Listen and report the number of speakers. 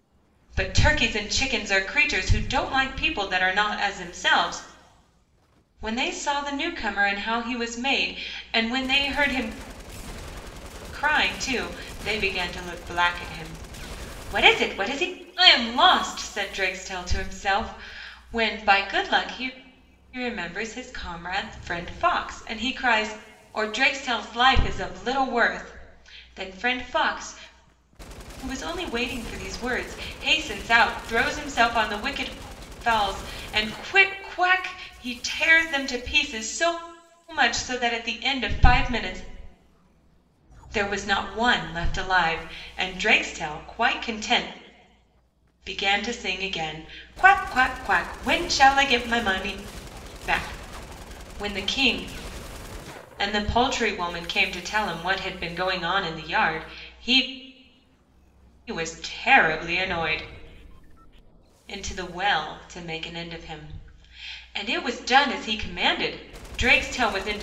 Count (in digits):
1